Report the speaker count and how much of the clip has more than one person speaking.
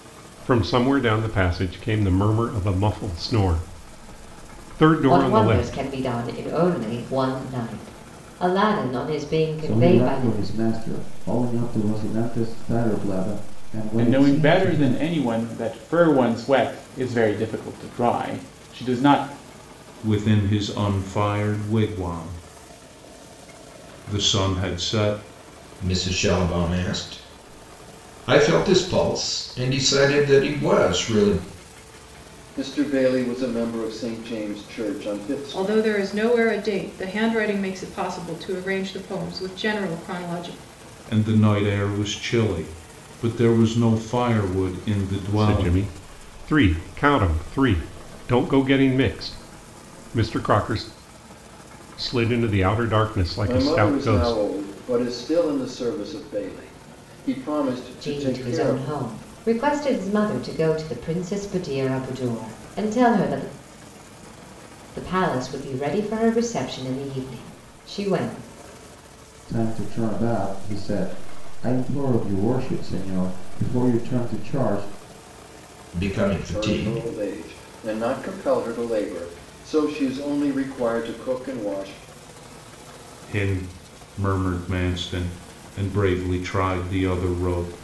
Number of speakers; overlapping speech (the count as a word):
eight, about 7%